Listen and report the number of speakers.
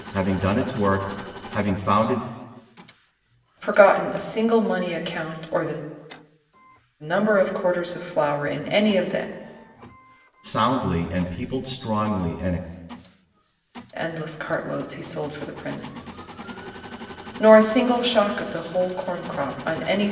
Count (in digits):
2